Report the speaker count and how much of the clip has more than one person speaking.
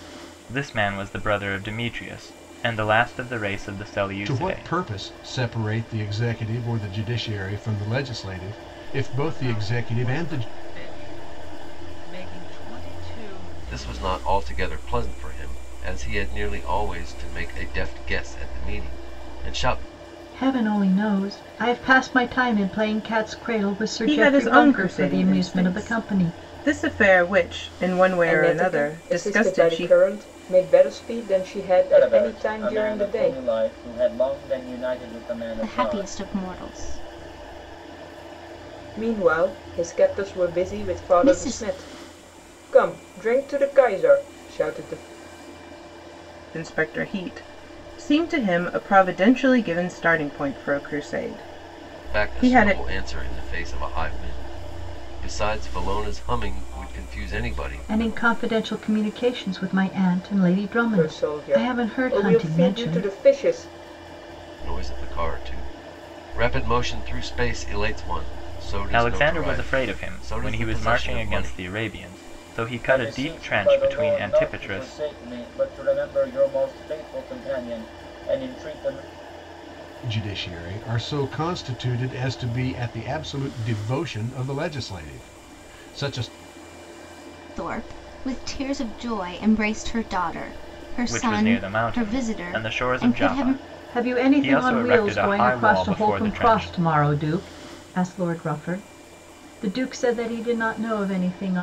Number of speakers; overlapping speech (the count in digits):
9, about 27%